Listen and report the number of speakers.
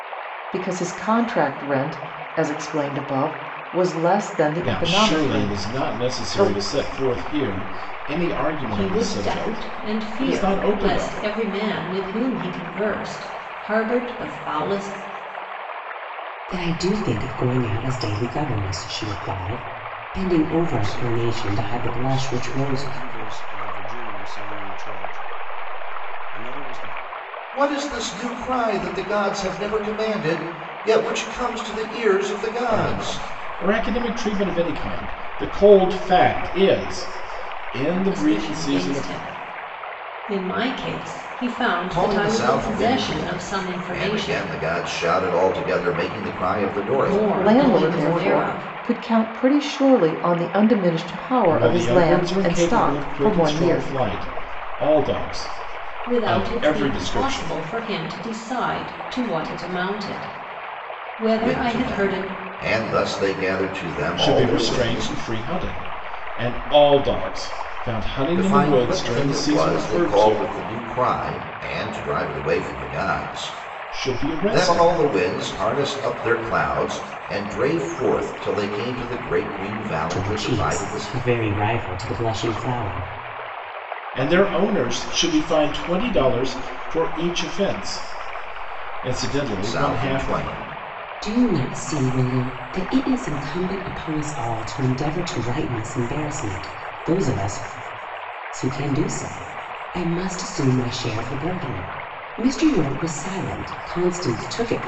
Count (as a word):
six